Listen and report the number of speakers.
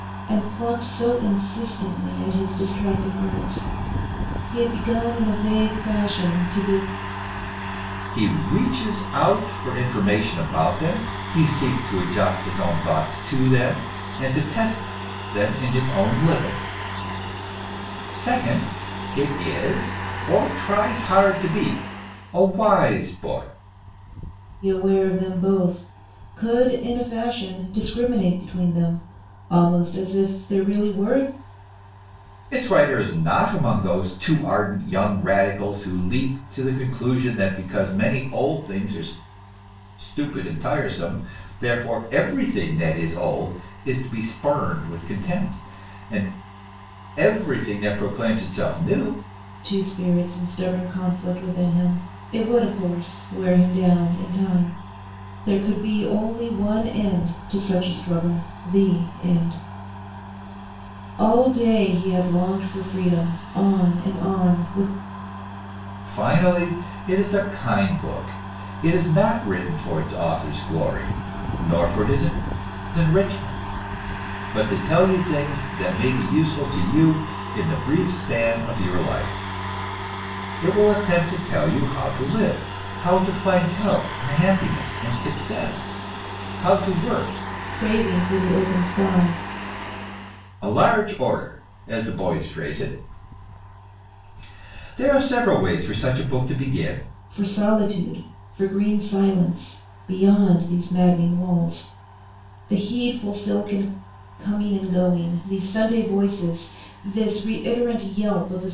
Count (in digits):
2